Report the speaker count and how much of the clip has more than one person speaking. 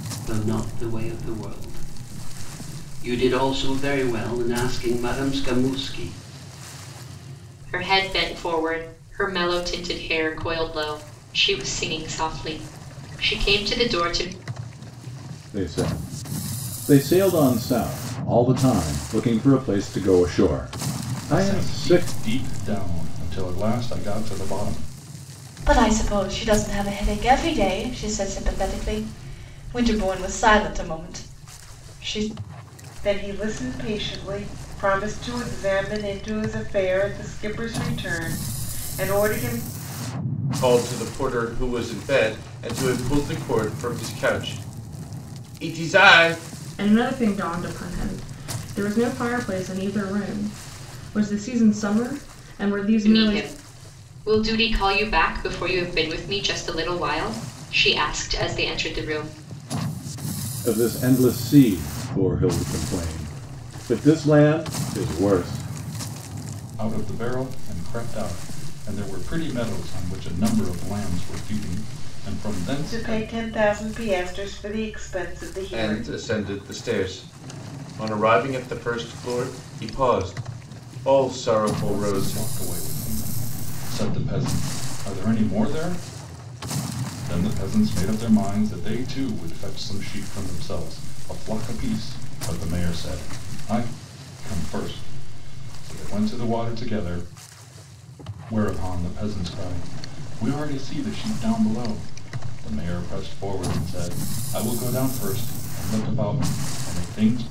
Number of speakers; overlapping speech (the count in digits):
8, about 3%